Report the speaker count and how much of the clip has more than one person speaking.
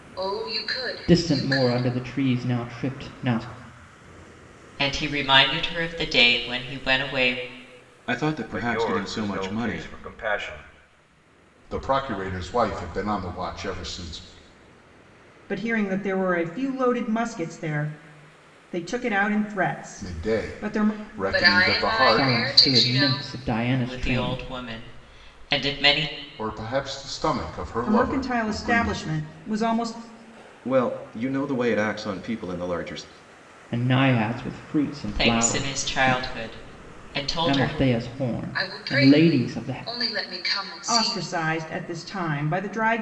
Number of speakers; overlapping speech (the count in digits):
7, about 23%